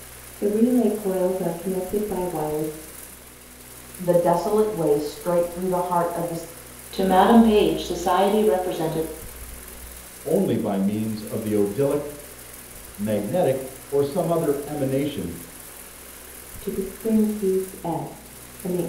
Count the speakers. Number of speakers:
four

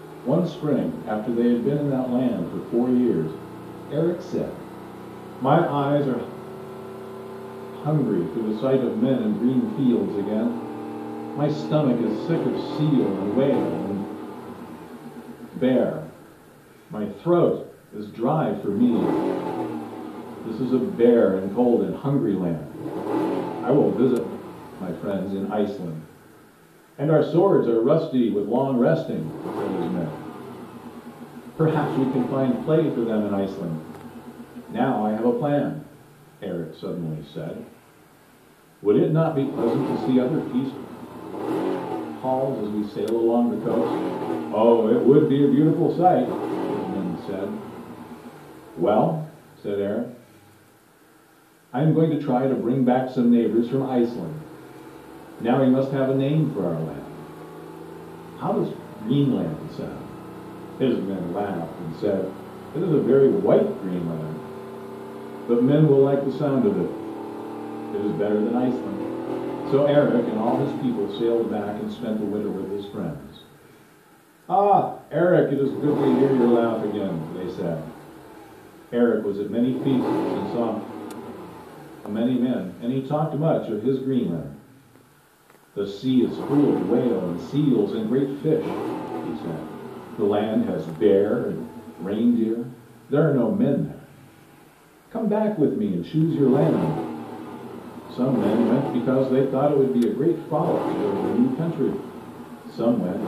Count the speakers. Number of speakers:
one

